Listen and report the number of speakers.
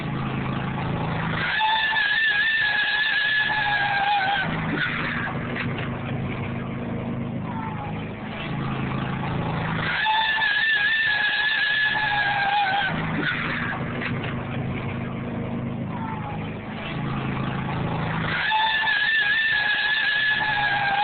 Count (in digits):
0